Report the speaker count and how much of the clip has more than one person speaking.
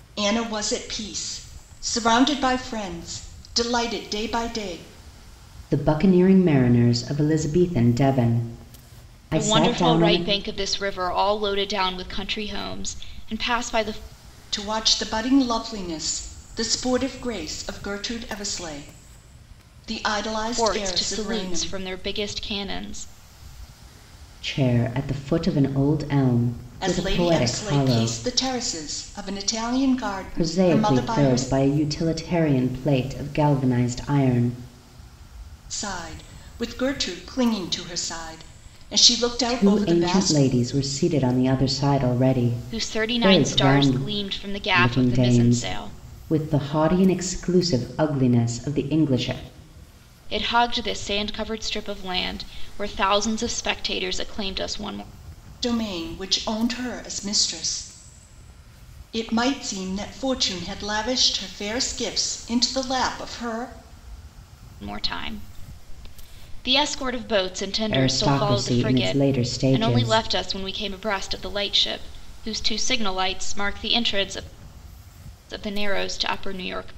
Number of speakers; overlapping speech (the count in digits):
3, about 14%